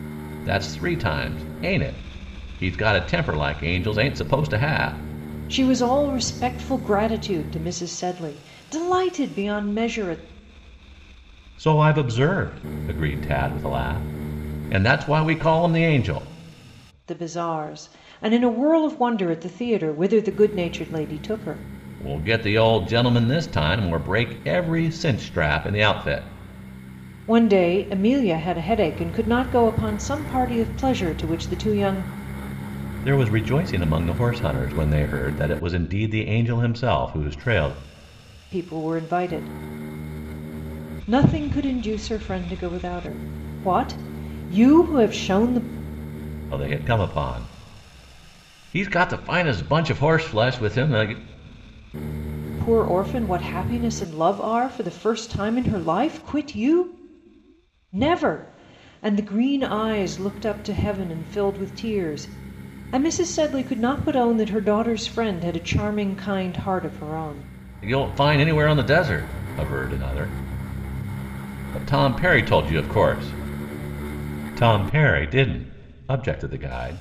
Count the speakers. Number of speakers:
two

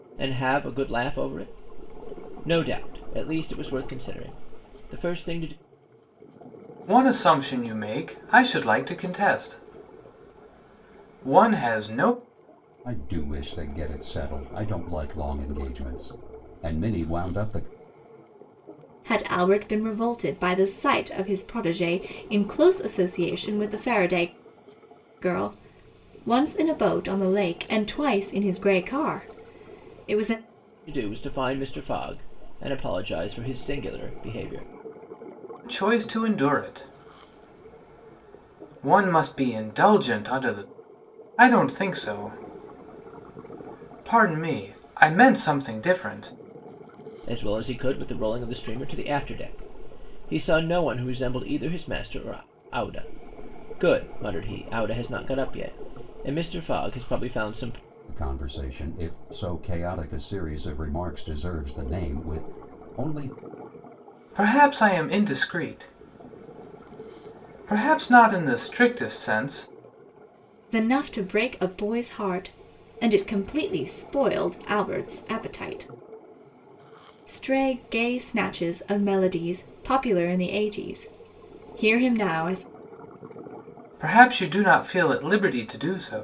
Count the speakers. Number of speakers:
four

